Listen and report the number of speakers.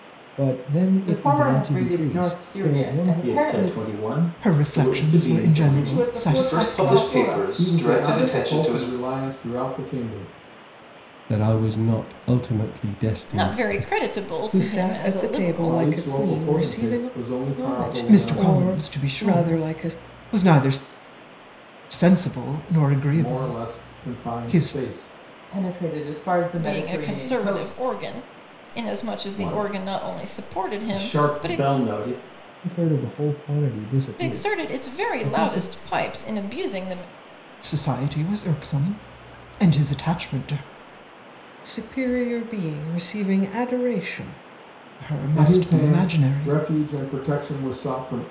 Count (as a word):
ten